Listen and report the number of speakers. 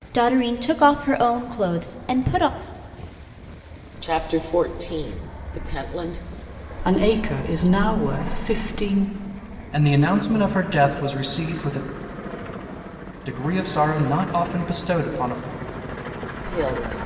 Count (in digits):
4